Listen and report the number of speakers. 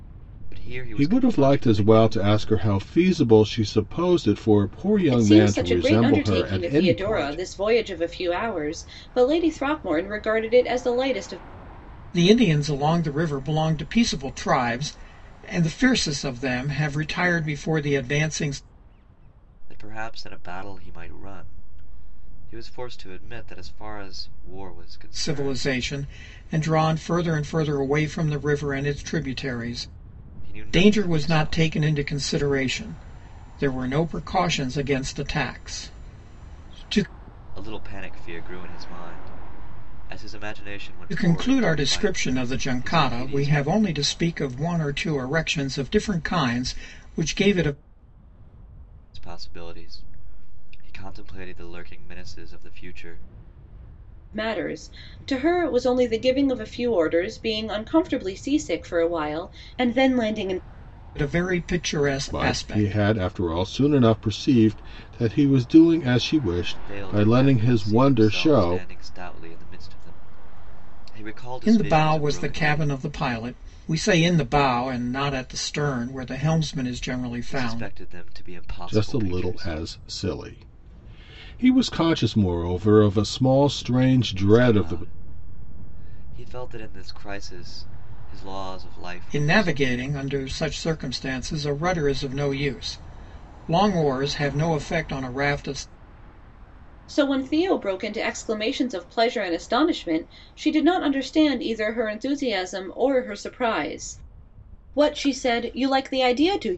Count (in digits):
4